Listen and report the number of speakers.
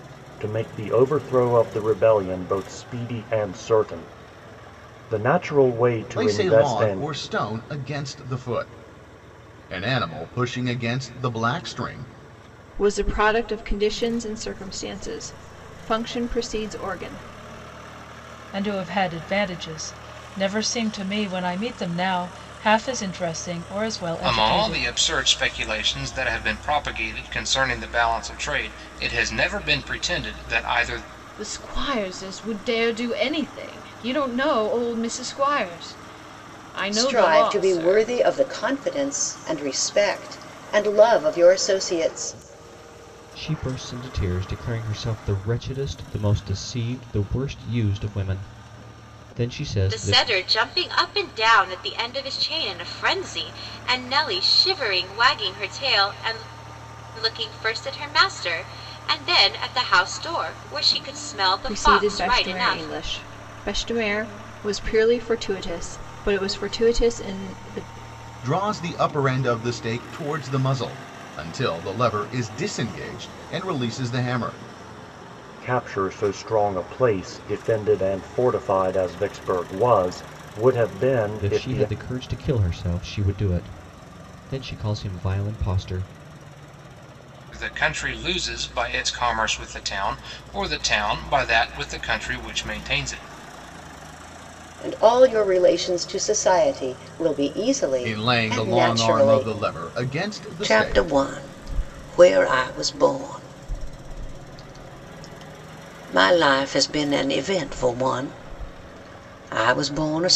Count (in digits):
9